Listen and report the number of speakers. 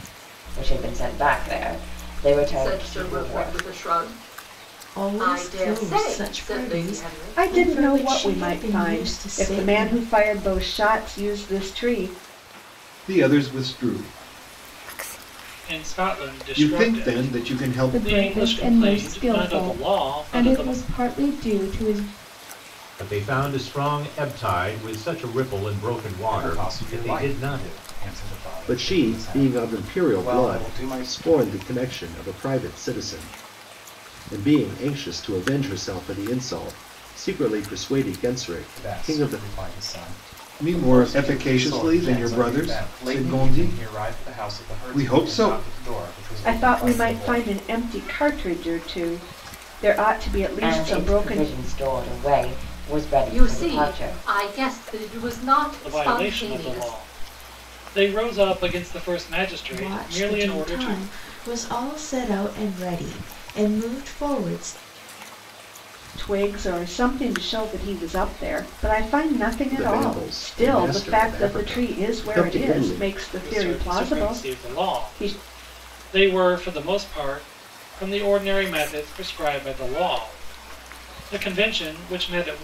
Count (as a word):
ten